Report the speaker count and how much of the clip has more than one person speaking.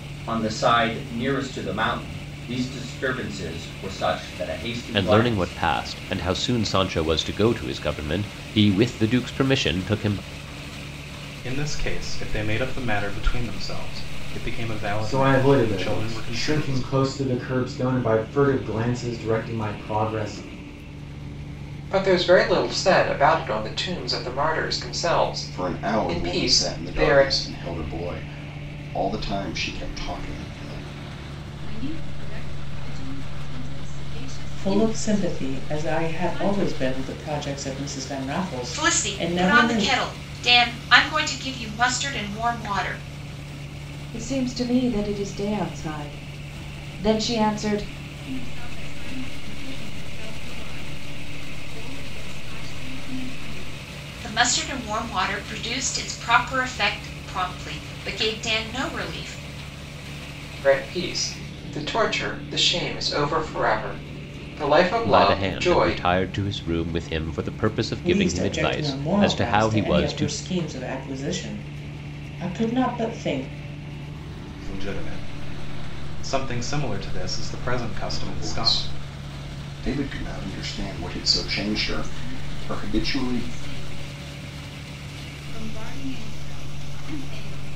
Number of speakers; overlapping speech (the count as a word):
ten, about 16%